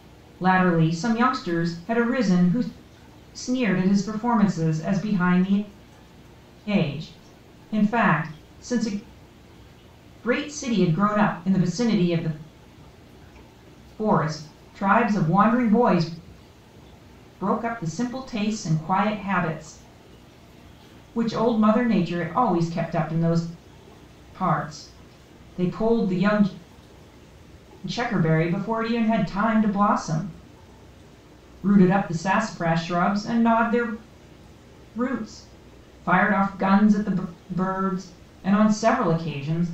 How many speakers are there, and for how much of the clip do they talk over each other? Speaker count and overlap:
one, no overlap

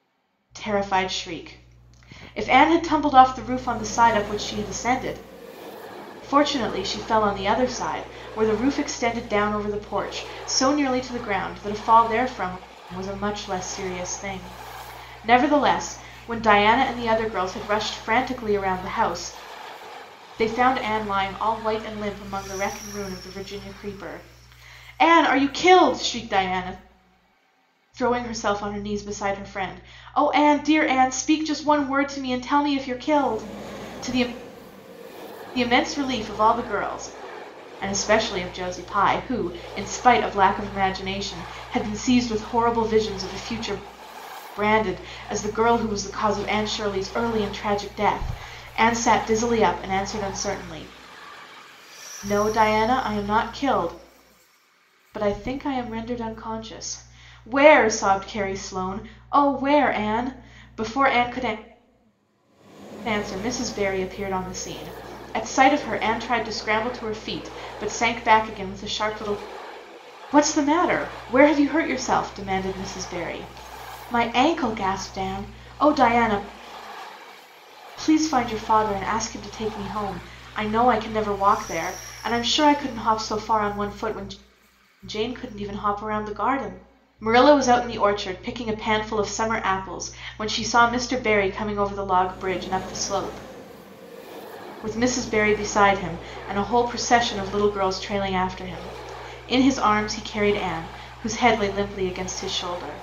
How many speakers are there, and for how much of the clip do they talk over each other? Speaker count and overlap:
one, no overlap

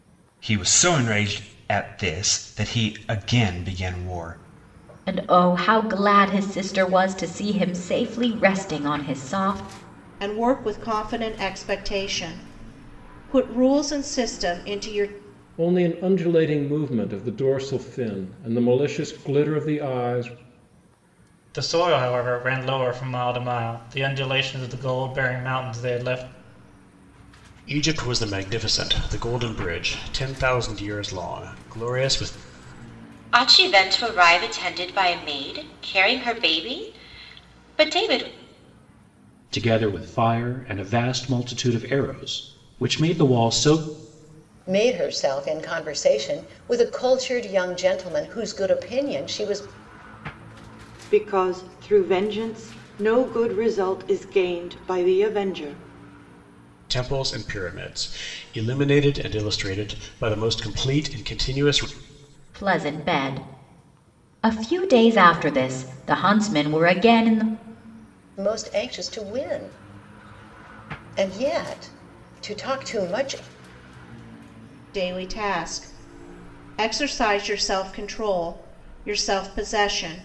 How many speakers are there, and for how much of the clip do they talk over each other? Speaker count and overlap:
ten, no overlap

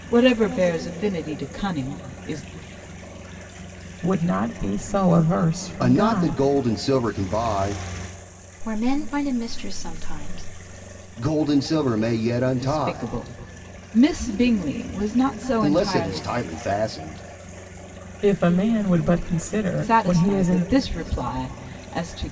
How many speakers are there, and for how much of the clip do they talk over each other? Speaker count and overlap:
four, about 13%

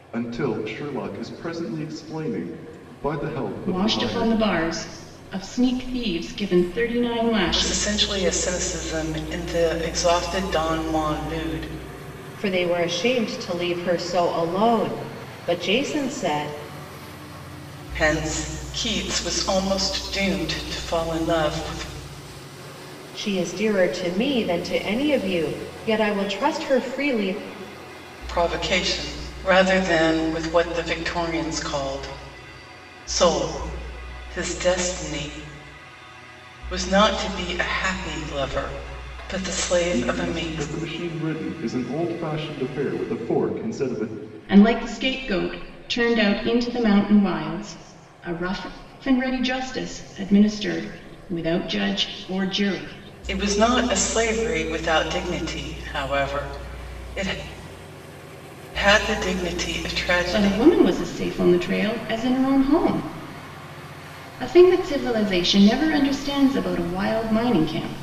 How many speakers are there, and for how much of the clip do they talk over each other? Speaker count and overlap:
four, about 3%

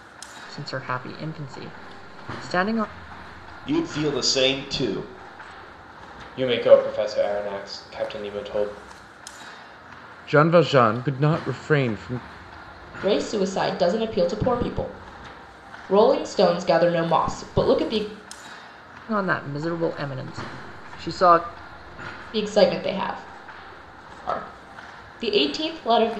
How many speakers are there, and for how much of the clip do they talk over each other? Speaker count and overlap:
five, no overlap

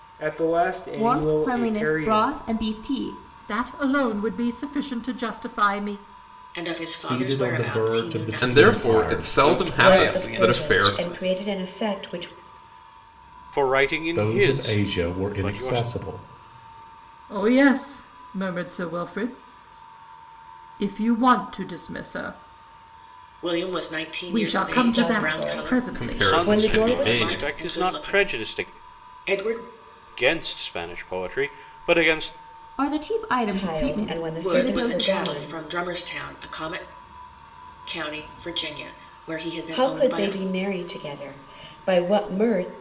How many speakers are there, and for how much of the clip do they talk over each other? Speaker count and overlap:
nine, about 34%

